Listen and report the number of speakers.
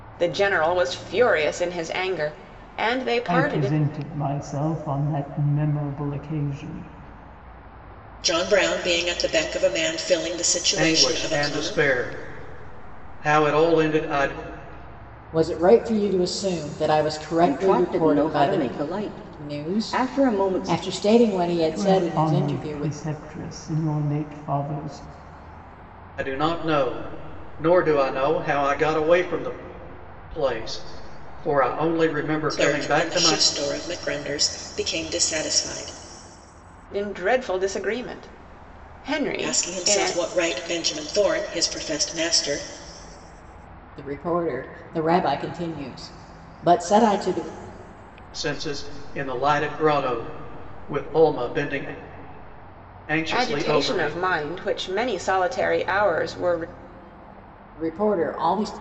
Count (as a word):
six